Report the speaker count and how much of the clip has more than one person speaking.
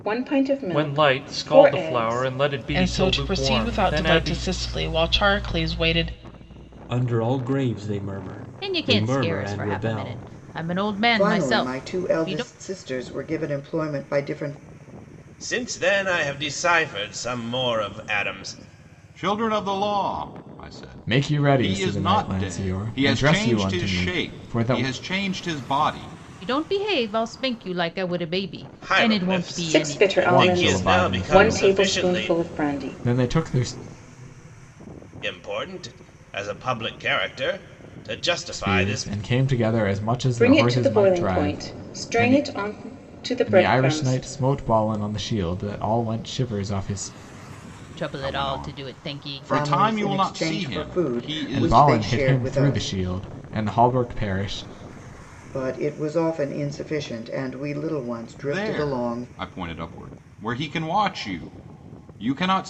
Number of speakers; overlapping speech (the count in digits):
9, about 37%